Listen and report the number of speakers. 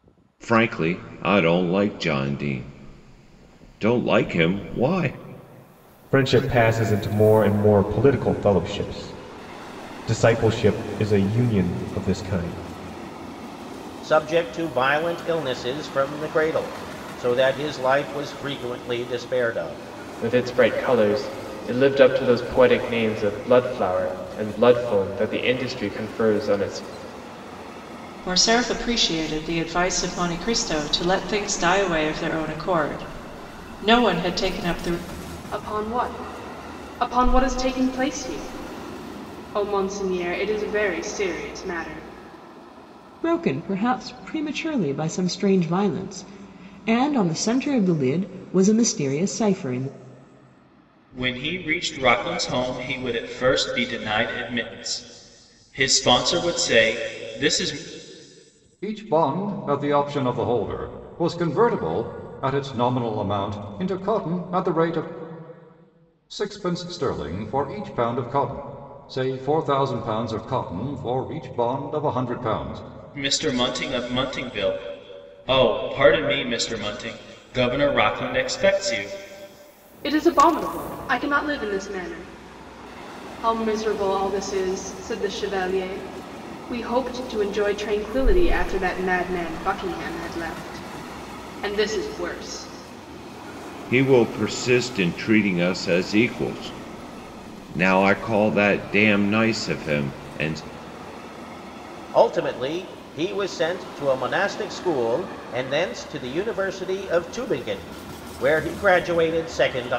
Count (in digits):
9